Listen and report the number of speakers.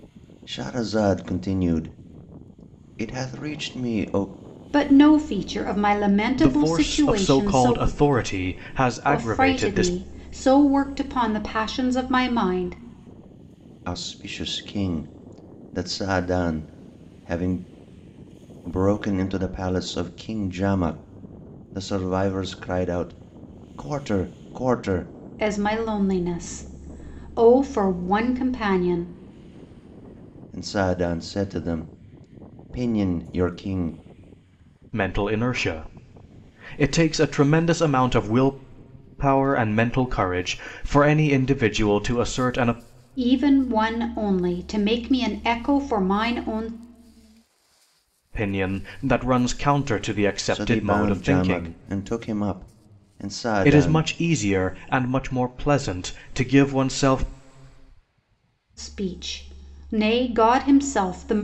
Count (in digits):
3